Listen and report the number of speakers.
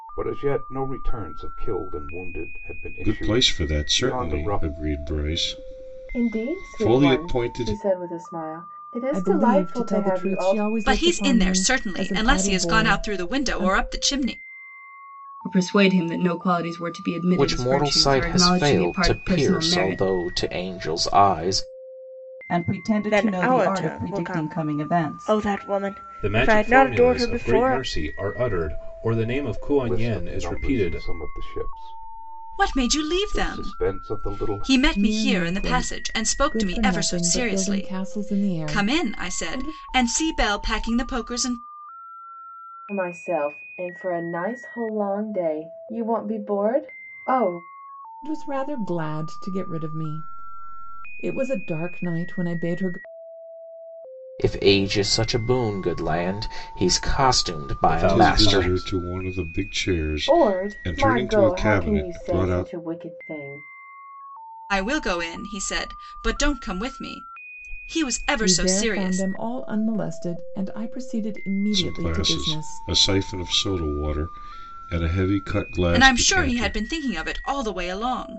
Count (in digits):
10